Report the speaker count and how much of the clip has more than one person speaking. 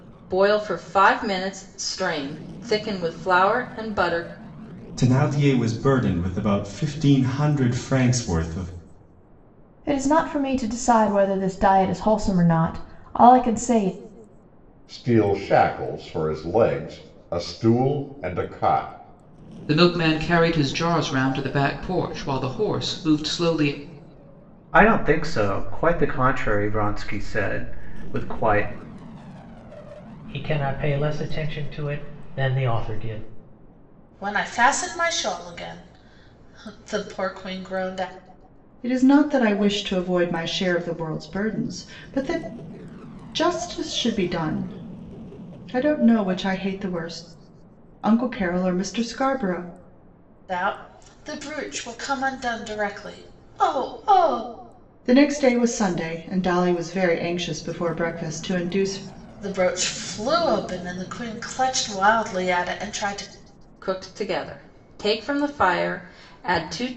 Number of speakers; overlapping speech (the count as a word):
nine, no overlap